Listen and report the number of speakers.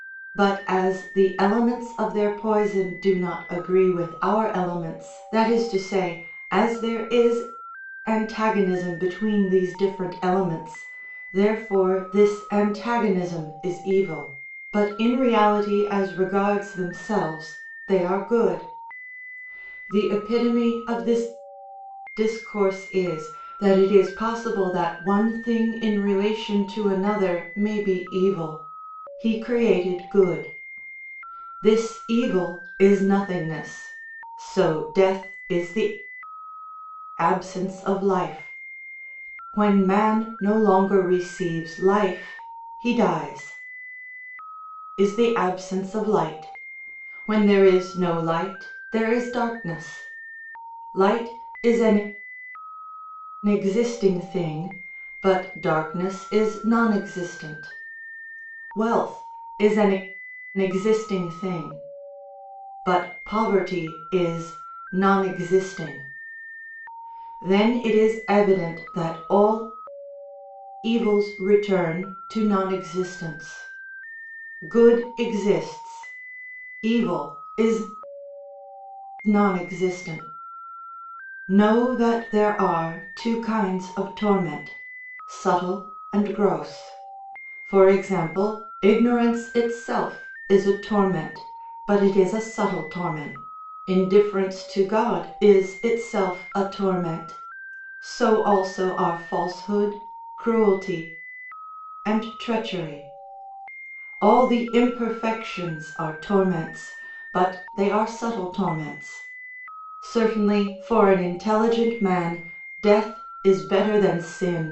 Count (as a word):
one